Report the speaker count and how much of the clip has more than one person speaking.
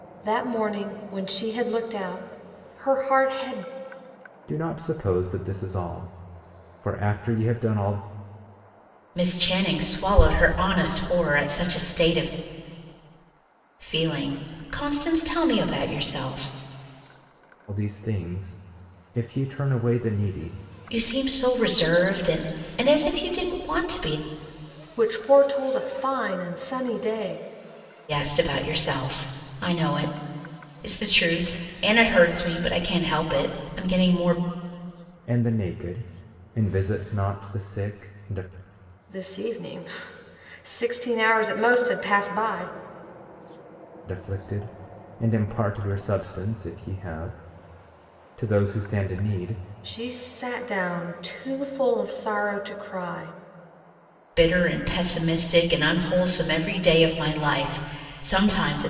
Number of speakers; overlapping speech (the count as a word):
three, no overlap